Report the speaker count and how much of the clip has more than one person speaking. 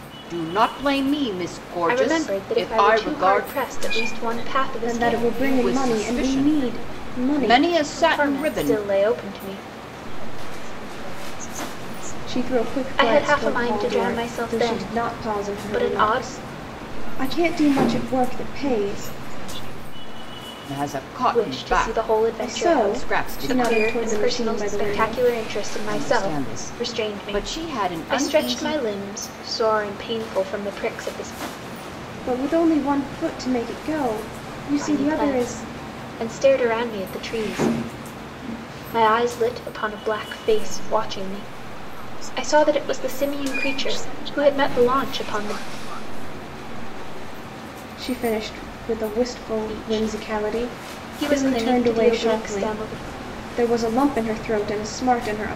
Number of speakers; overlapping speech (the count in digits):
4, about 50%